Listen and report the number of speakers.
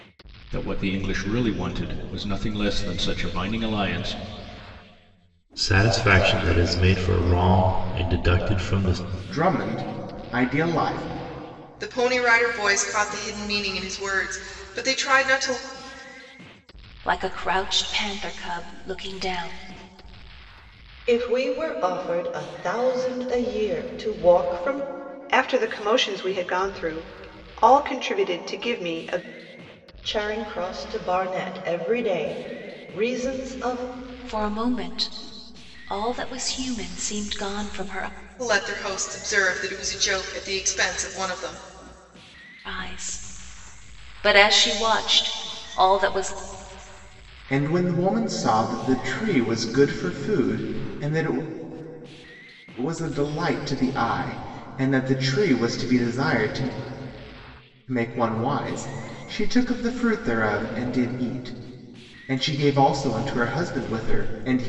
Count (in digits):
7